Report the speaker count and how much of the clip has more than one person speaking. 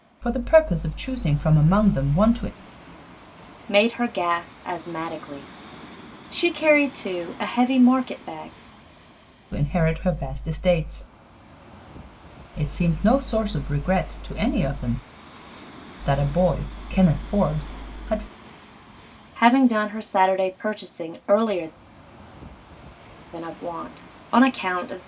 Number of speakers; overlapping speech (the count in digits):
2, no overlap